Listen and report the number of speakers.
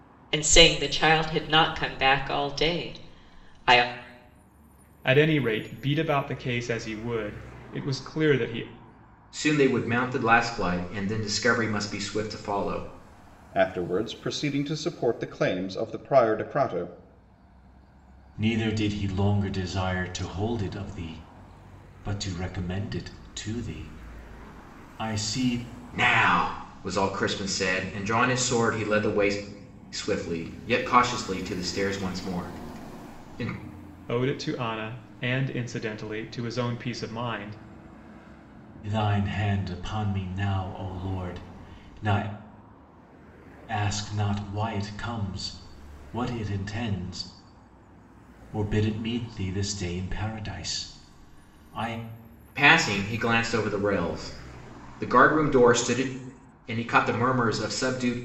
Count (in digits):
5